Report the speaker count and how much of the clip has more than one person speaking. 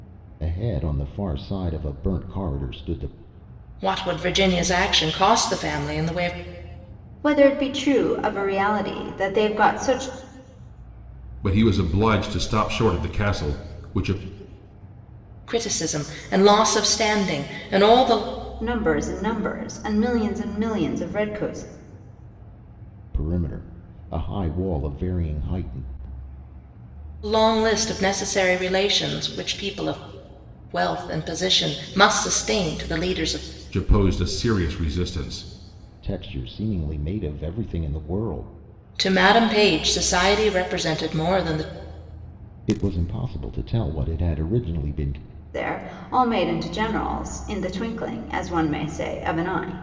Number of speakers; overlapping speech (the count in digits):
4, no overlap